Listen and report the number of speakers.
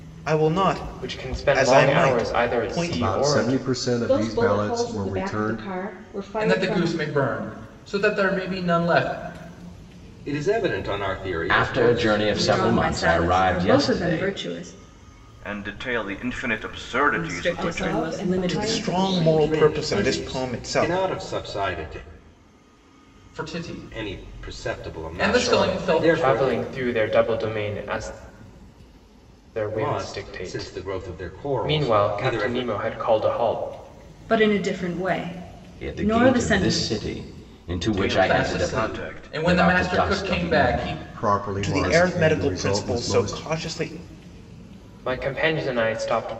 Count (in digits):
9